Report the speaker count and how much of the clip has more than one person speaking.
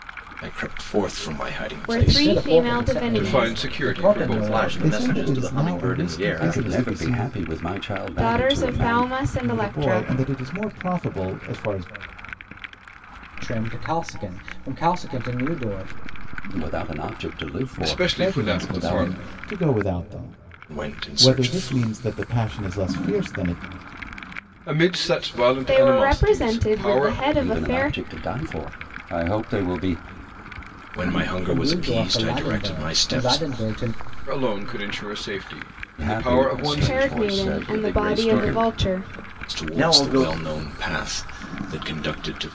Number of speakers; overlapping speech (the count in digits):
7, about 41%